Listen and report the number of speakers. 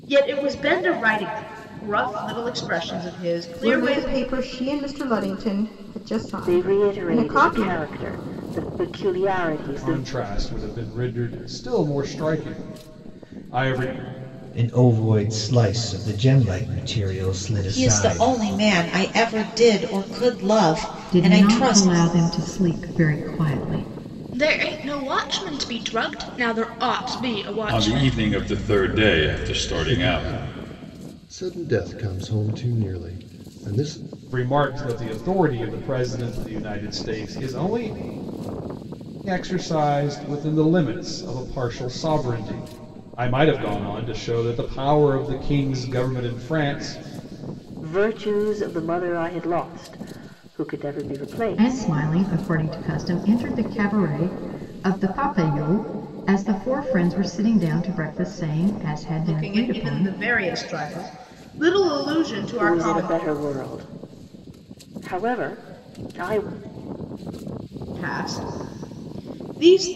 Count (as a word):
ten